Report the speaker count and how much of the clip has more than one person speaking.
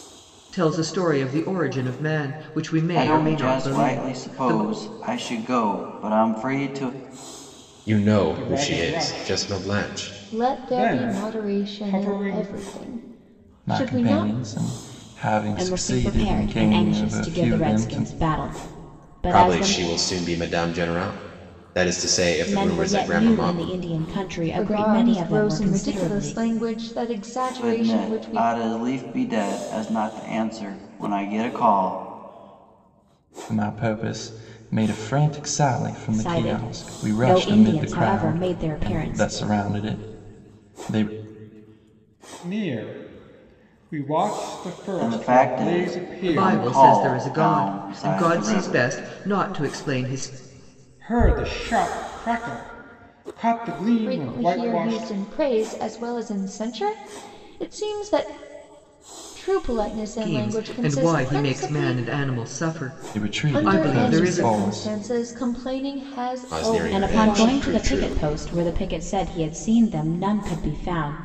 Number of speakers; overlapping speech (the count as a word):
seven, about 38%